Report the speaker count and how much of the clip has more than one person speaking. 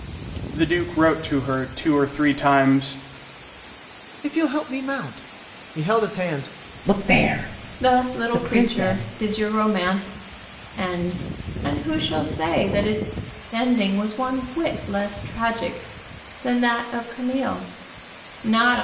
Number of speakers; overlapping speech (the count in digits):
4, about 7%